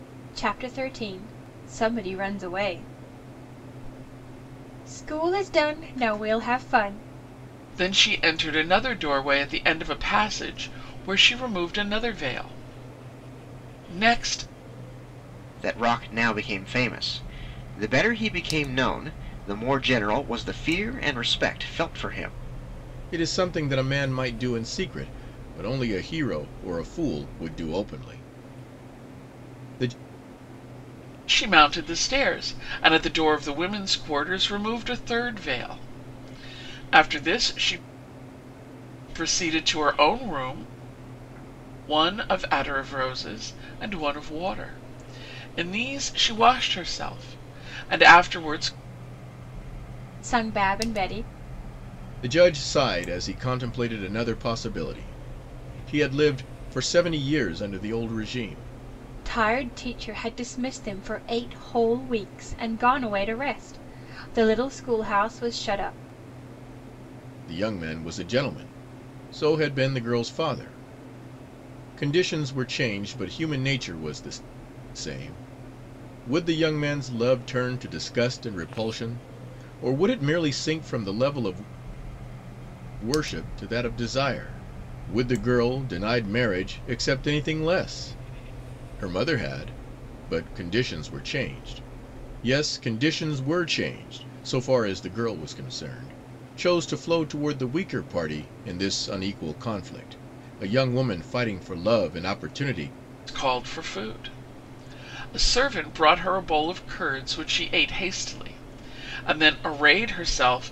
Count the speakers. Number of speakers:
4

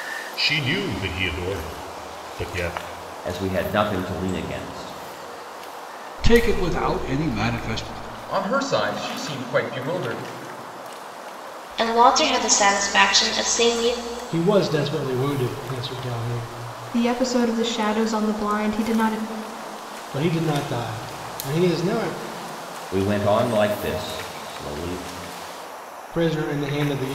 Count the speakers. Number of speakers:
7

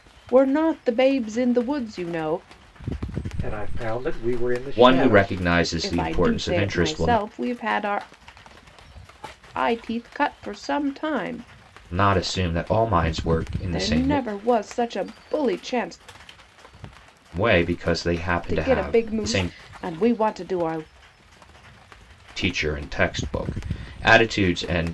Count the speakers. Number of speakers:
3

